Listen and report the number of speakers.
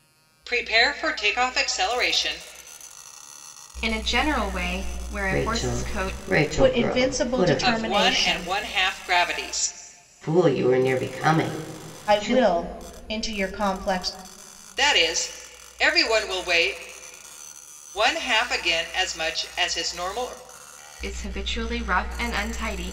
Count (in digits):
4